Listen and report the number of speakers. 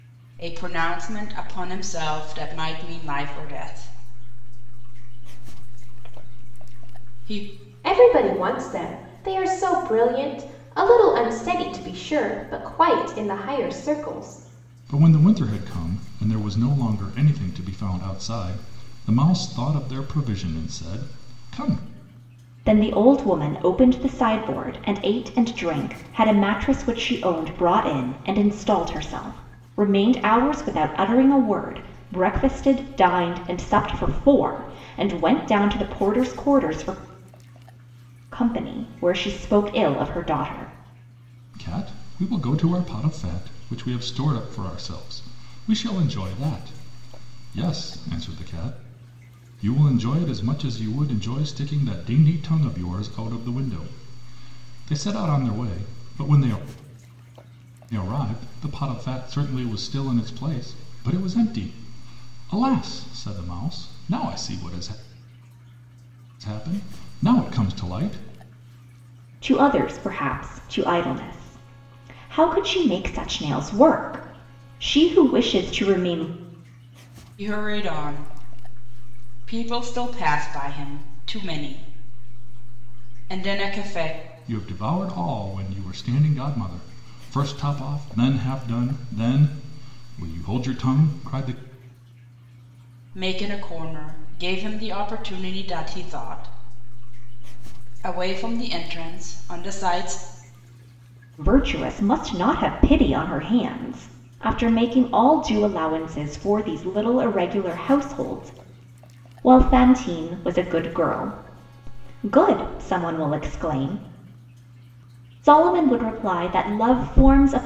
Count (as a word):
four